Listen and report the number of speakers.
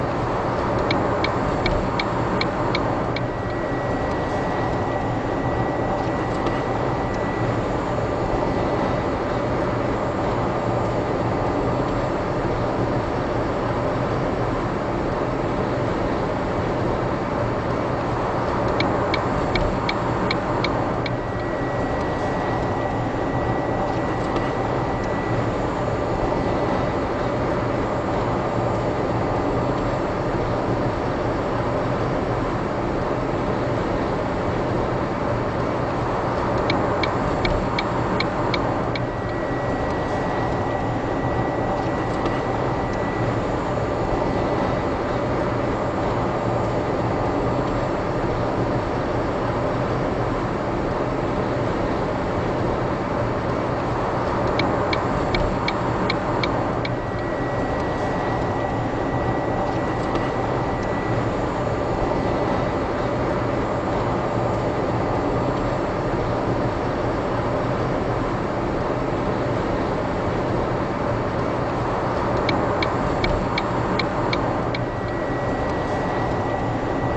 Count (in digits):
0